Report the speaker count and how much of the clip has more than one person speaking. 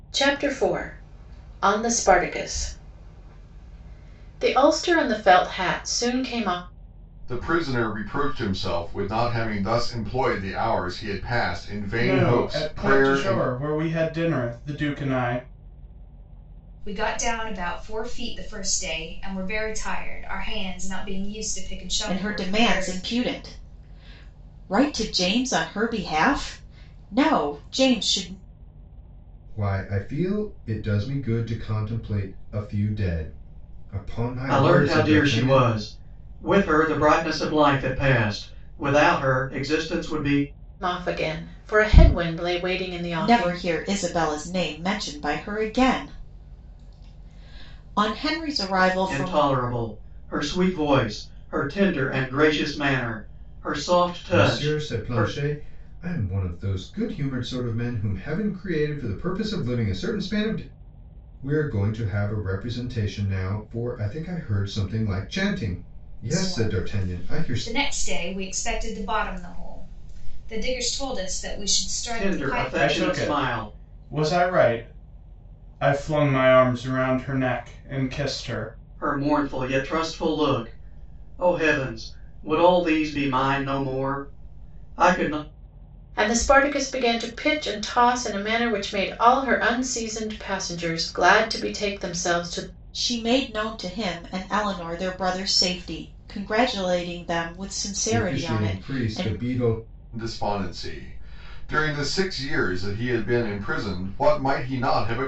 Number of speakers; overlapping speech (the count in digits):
7, about 9%